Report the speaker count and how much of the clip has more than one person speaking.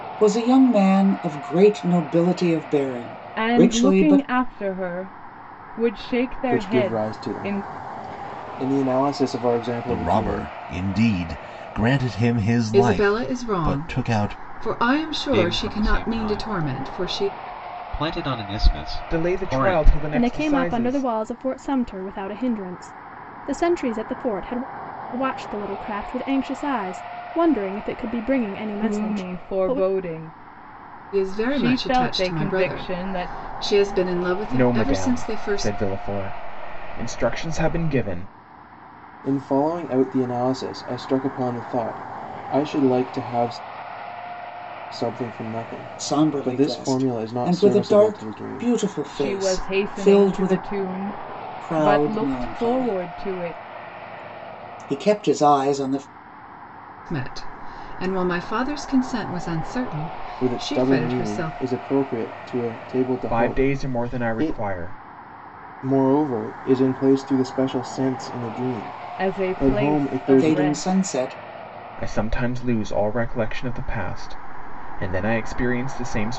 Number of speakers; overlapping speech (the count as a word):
eight, about 32%